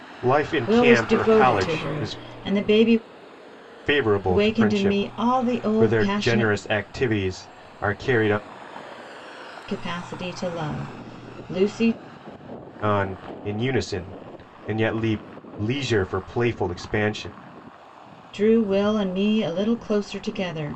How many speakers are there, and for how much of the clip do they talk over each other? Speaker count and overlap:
2, about 19%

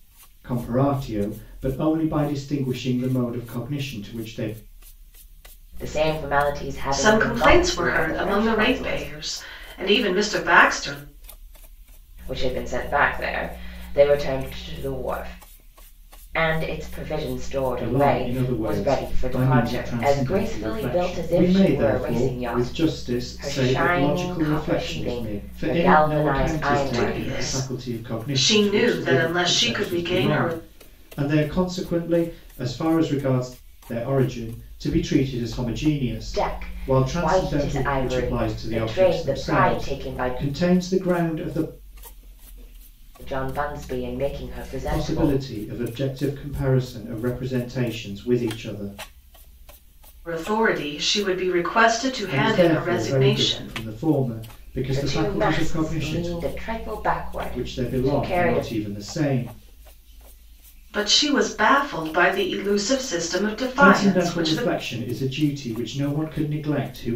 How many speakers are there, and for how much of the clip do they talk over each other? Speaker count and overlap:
3, about 37%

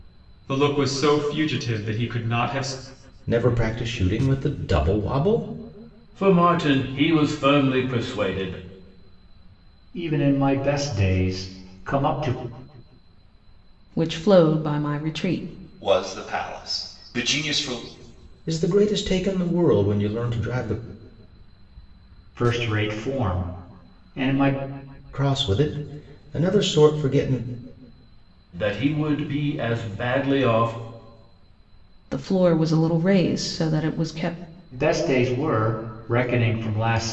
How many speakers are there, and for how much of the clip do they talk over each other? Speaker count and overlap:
6, no overlap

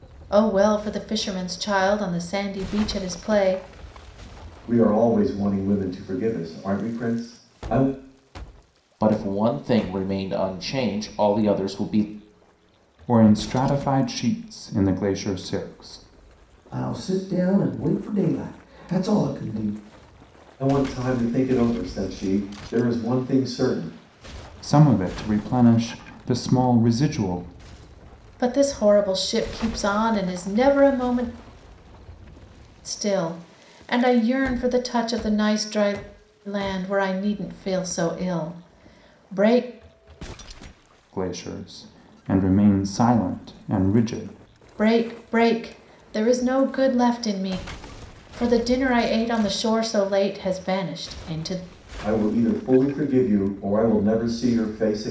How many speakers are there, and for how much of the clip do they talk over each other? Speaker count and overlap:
5, no overlap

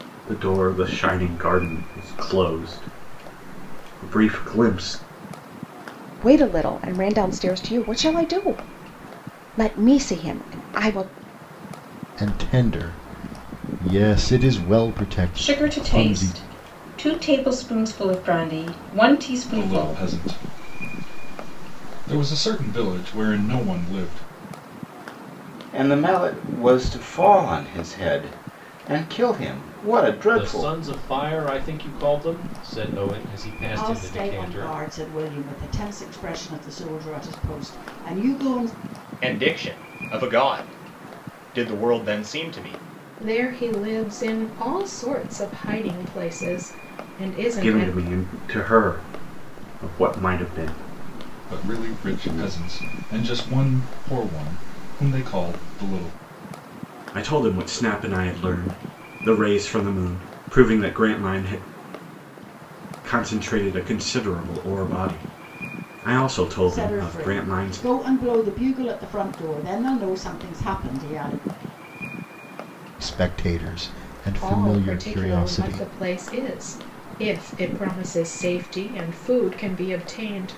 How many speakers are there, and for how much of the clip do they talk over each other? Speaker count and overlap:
10, about 9%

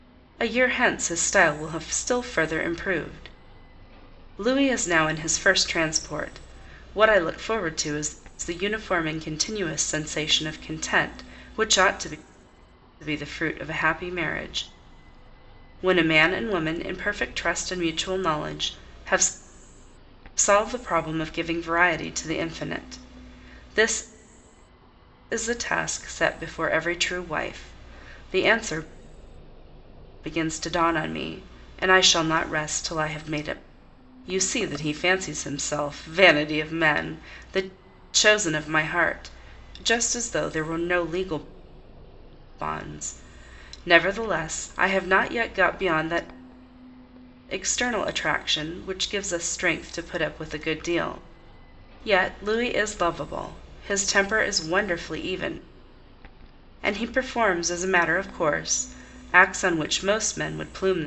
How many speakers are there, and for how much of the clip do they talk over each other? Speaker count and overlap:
1, no overlap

